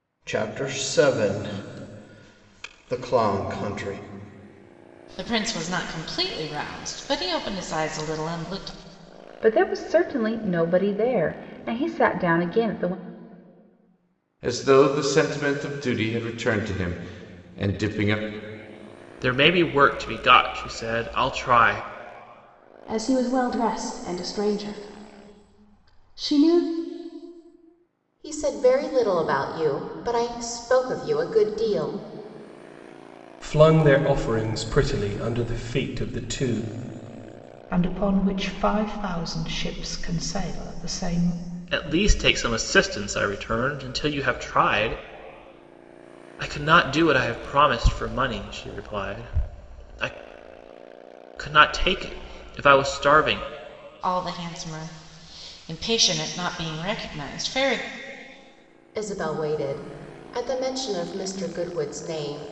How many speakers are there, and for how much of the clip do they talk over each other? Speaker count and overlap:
9, no overlap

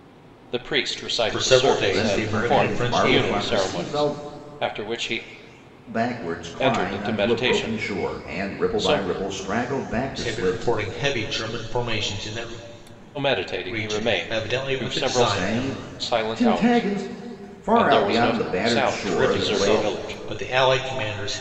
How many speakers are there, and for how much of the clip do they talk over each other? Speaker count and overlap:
3, about 54%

